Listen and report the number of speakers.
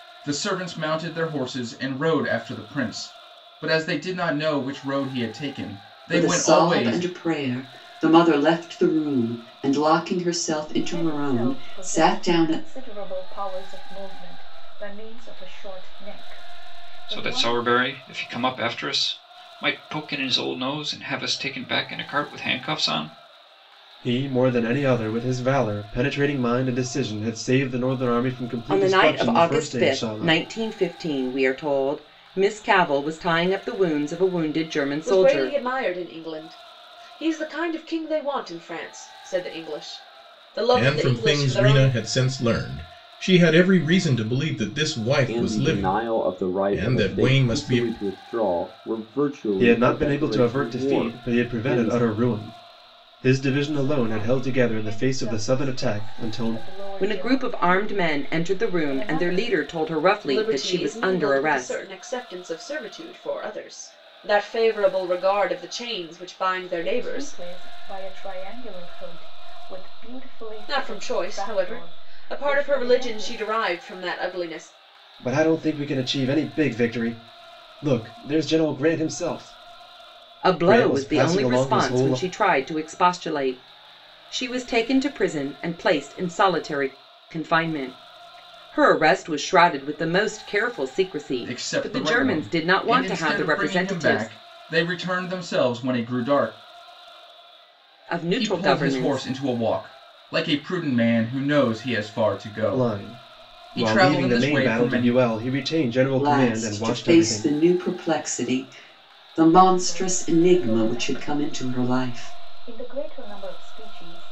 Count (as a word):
nine